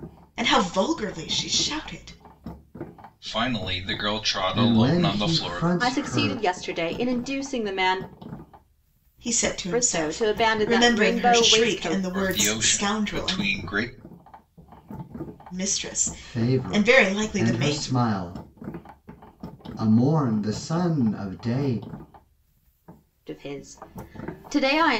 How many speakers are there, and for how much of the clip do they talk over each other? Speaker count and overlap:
four, about 29%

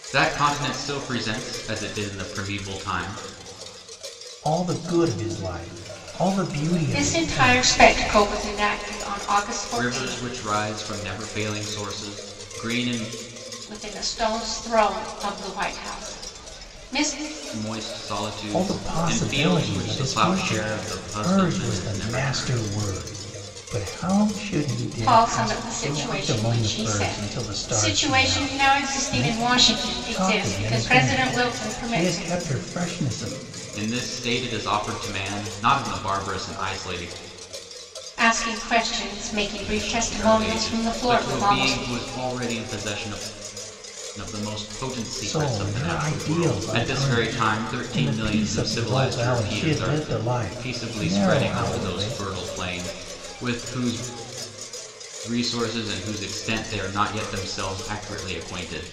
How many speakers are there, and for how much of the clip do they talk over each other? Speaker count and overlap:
three, about 36%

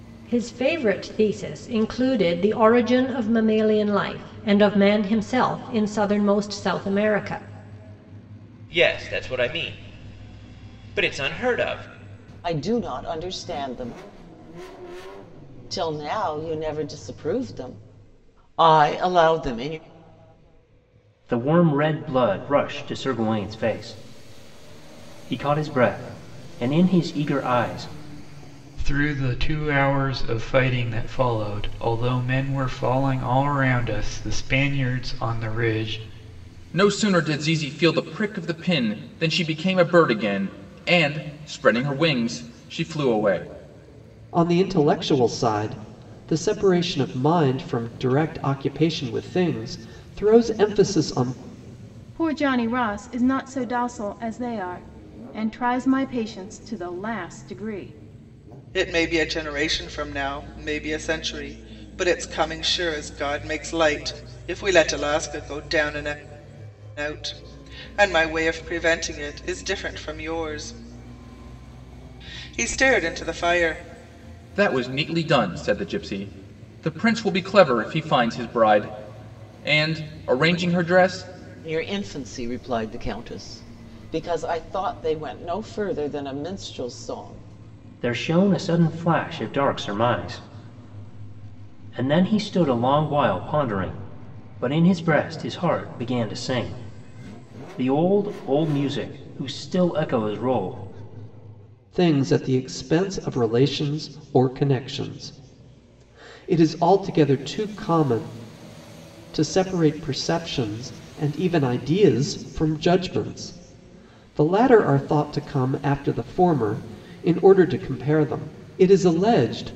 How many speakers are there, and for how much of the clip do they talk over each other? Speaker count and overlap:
nine, no overlap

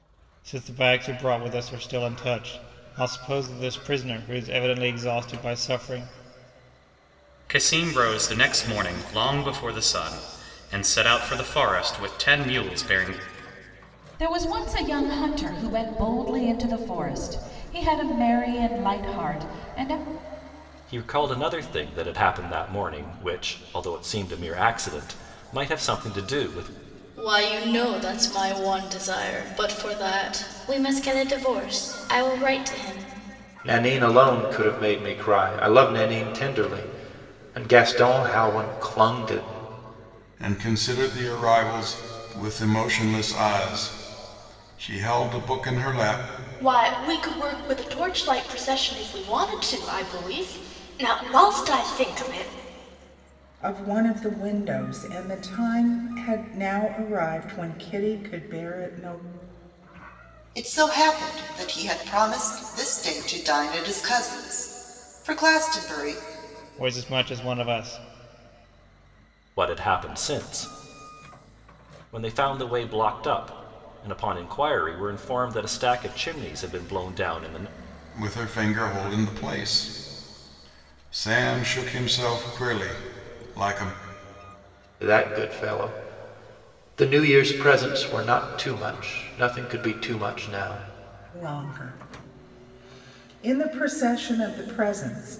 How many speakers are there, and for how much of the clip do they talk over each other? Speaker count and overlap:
ten, no overlap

